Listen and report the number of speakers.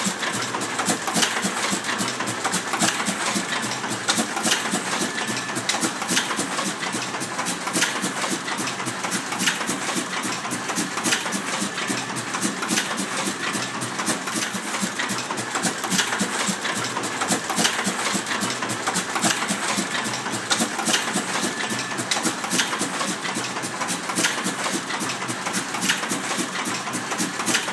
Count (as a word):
zero